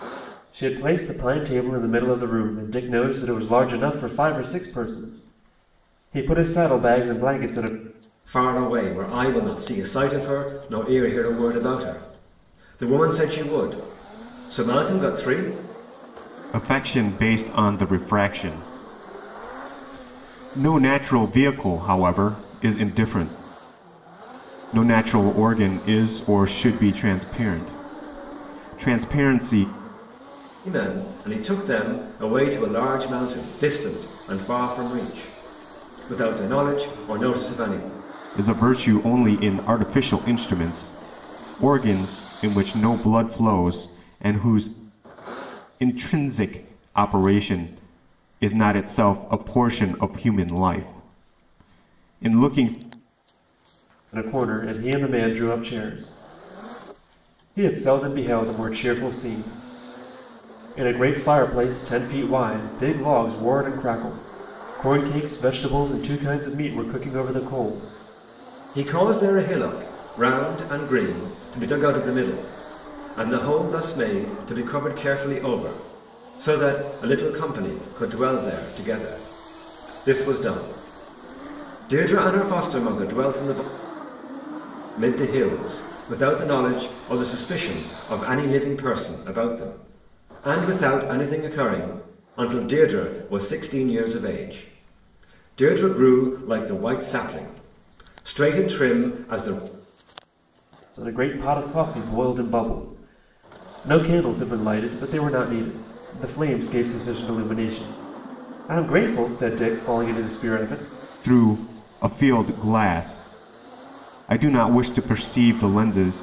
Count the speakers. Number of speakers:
3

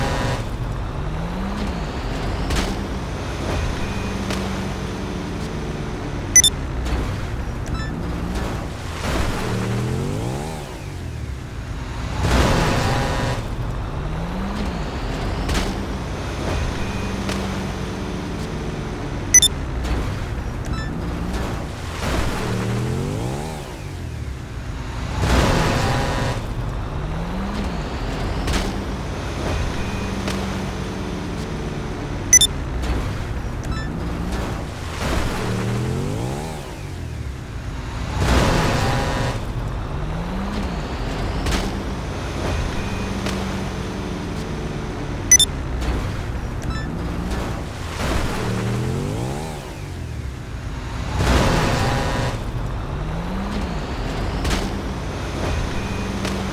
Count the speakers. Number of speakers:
0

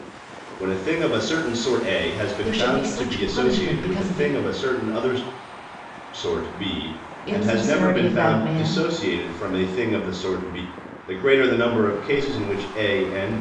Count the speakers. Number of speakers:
2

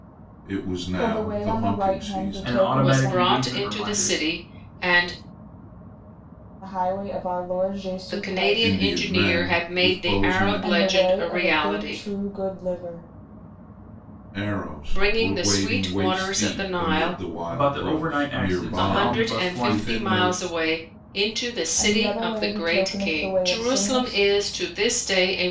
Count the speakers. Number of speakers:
4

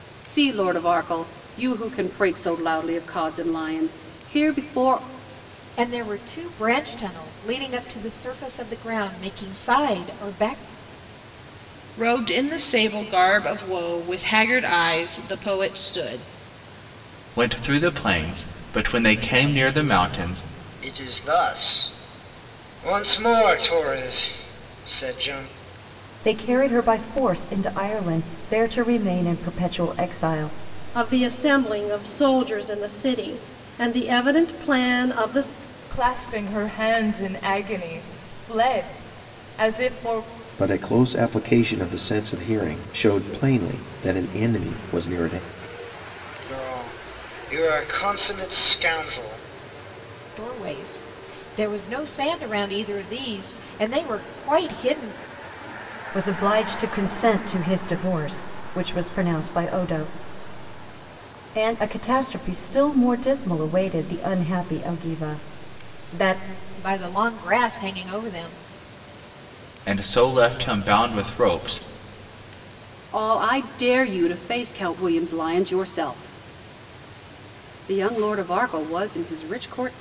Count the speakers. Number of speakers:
9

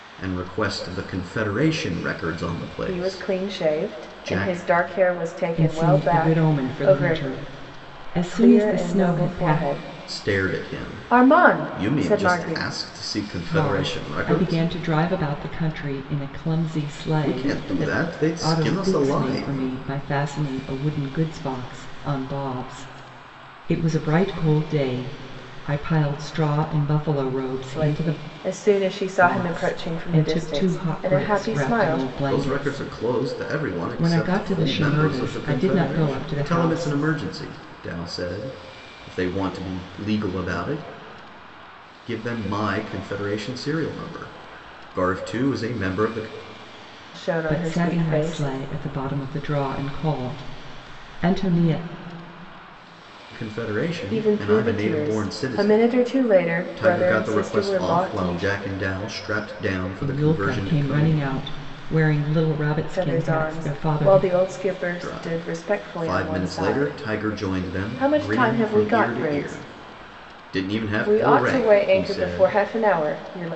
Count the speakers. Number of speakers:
3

